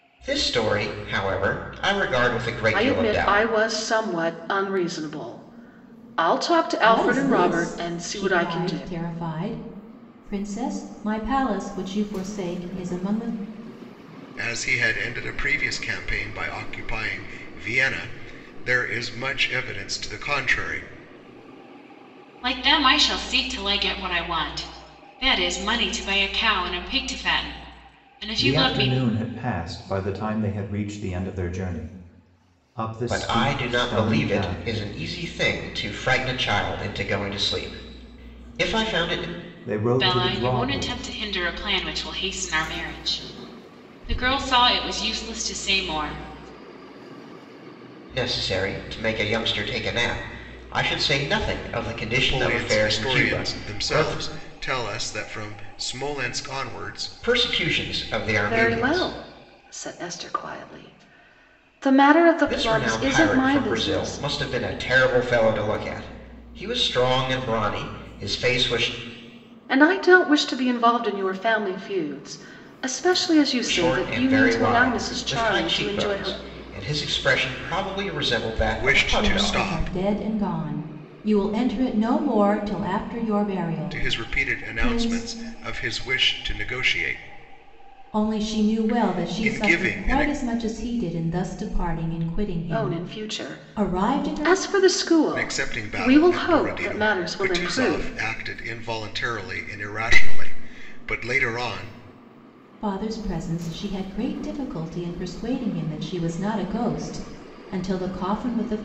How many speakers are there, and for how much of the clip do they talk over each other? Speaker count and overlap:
six, about 23%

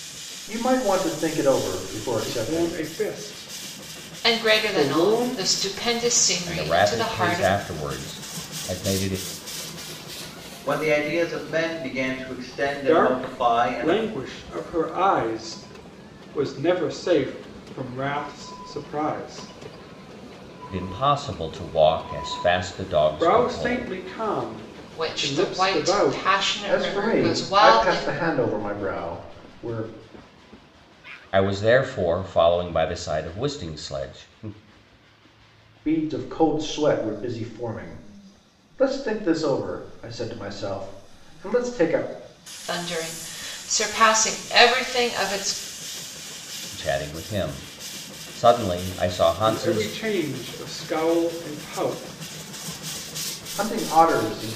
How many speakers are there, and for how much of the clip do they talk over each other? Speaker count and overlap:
five, about 15%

